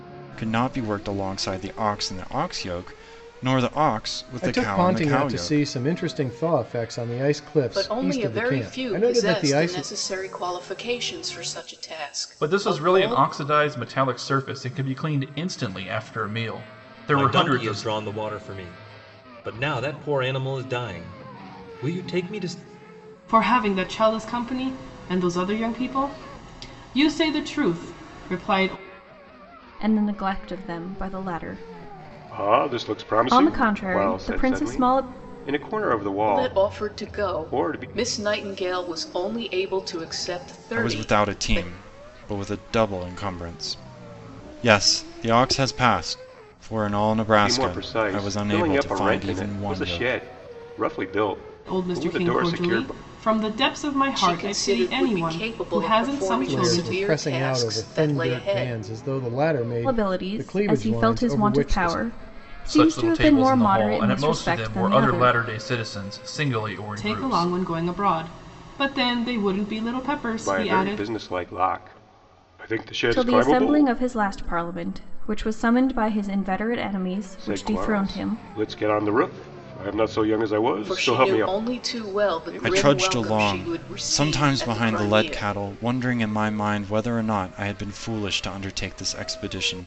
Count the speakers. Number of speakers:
8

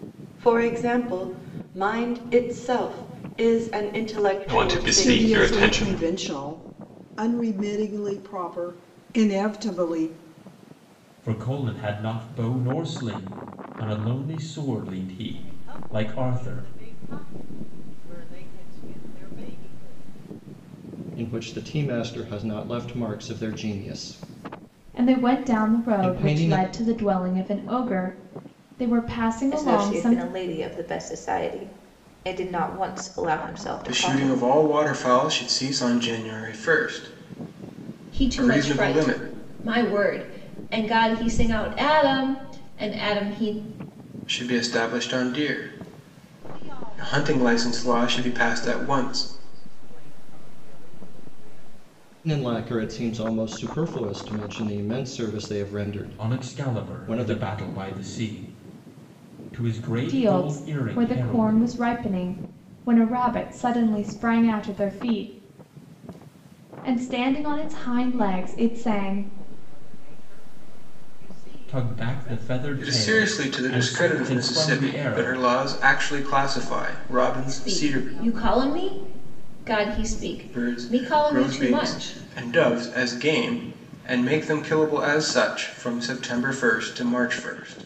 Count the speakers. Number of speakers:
10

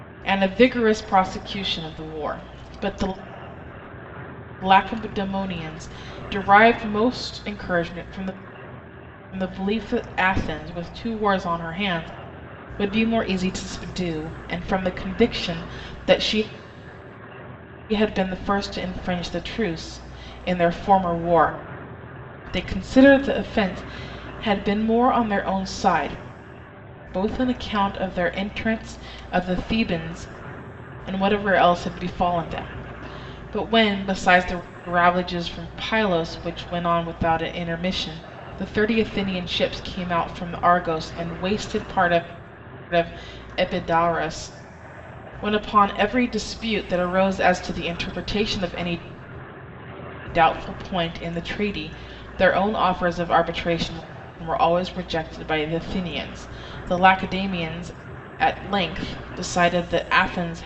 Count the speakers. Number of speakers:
1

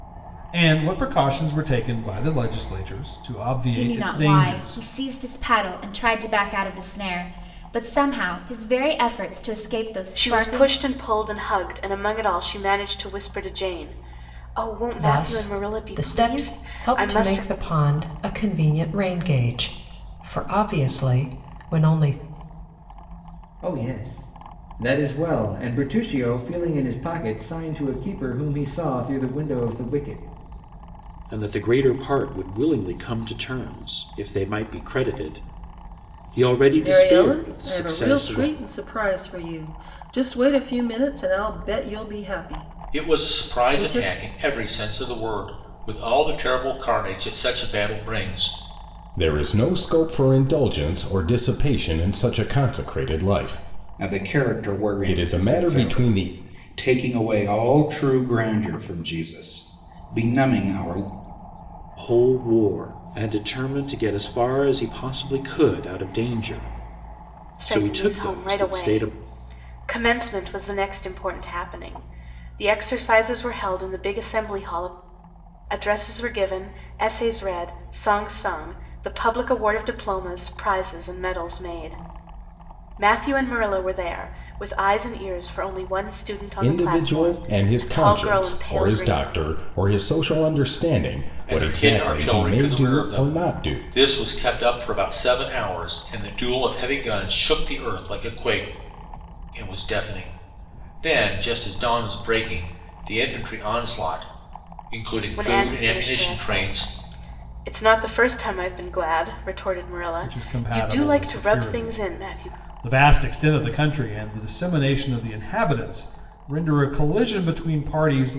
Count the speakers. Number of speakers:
10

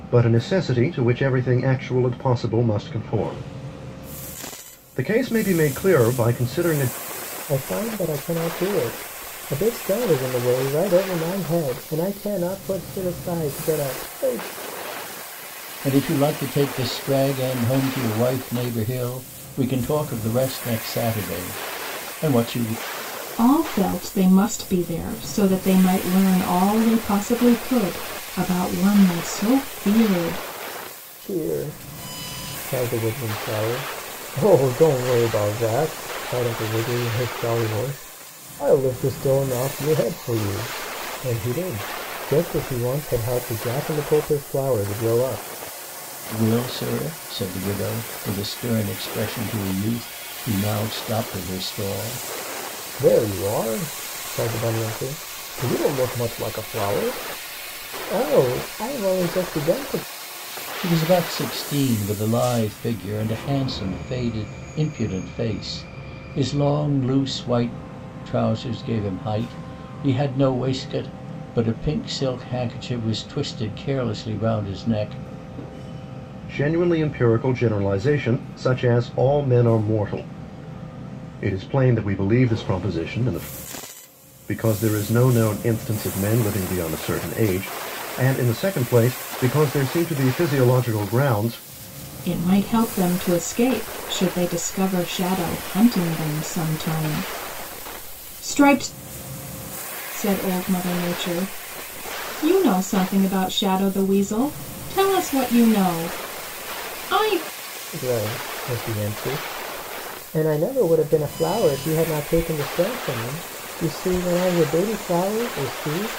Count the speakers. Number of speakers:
4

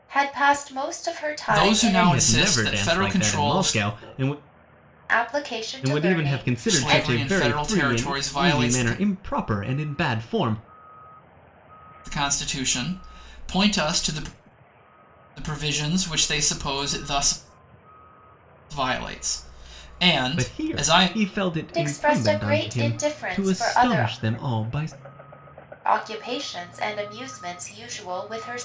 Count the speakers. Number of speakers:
3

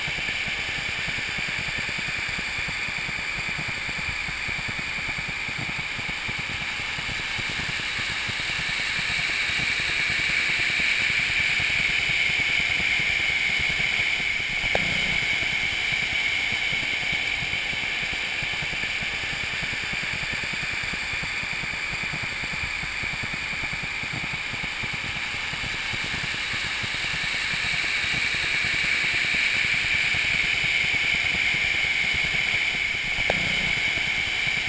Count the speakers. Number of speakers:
0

